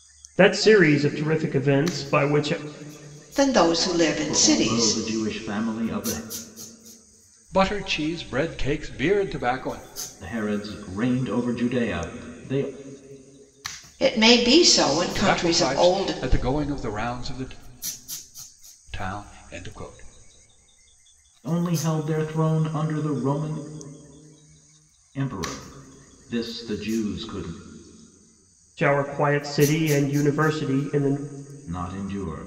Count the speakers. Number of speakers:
4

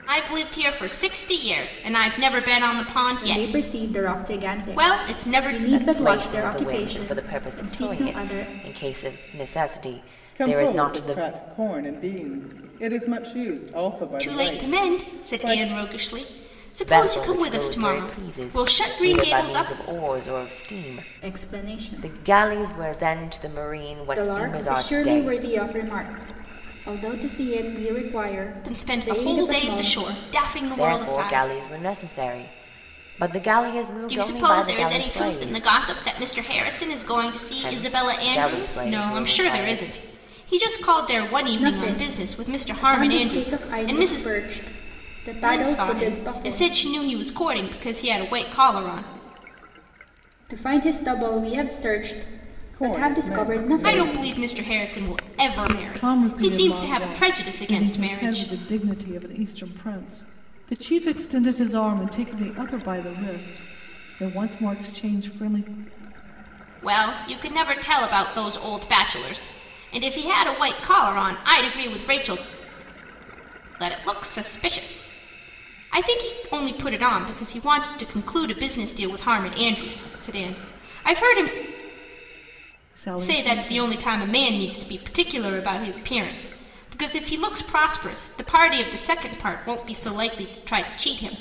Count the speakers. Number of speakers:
4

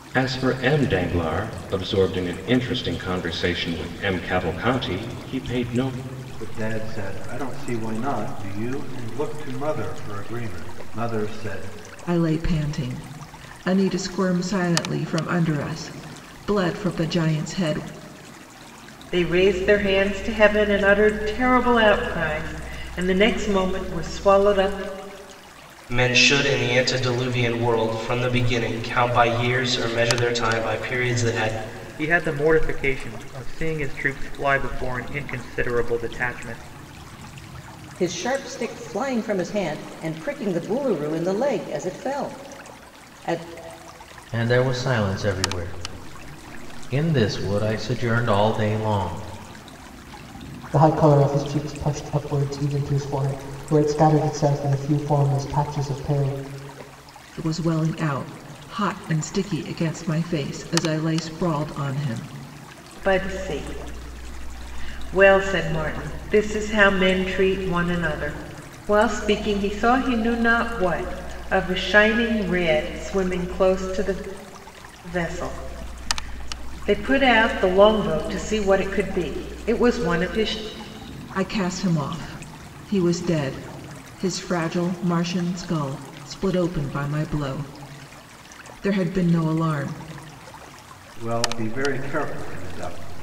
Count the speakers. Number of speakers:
9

